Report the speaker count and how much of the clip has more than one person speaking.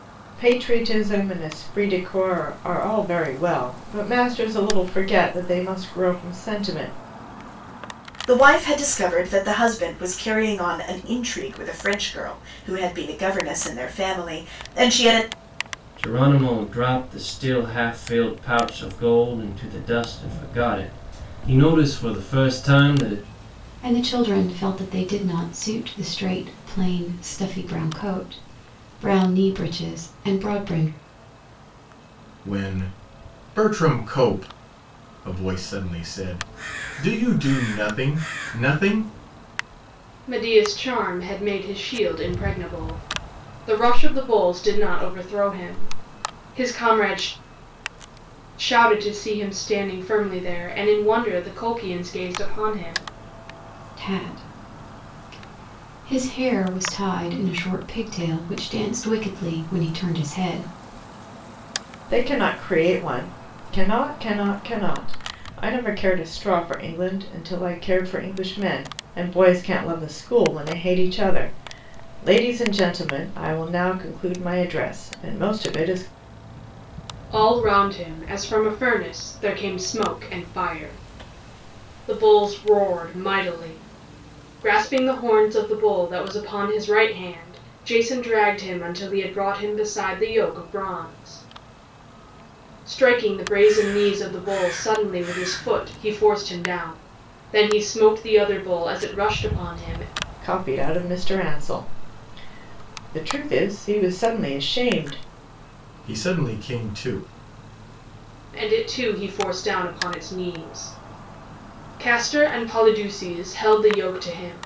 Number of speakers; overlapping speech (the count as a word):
six, no overlap